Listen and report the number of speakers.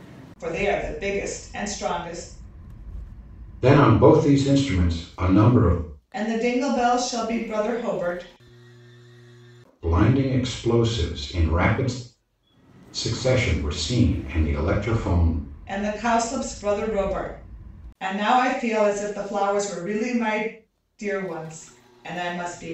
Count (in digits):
2